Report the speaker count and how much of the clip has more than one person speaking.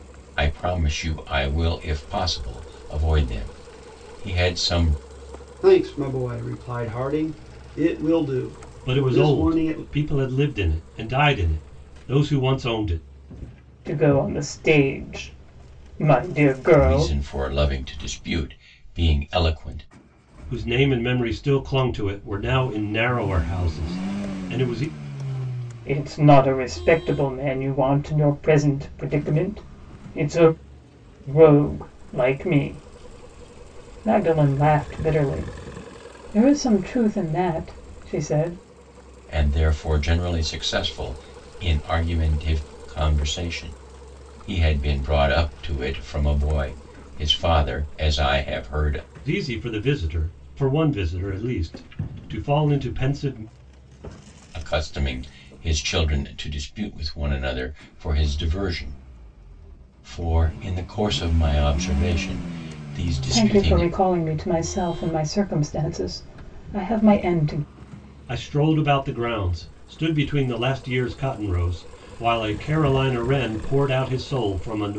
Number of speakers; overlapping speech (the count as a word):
four, about 3%